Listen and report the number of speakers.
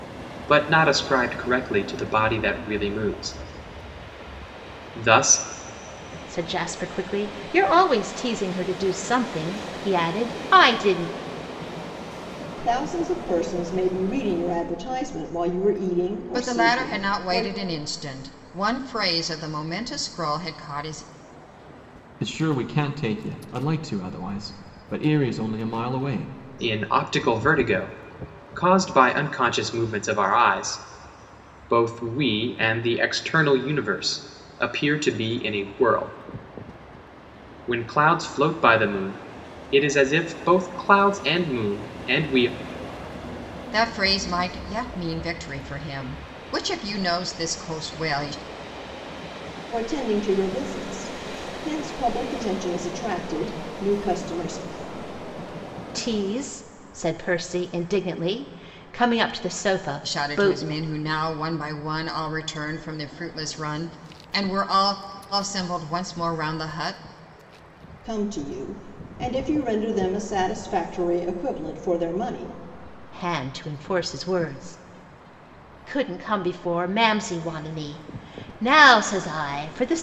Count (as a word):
five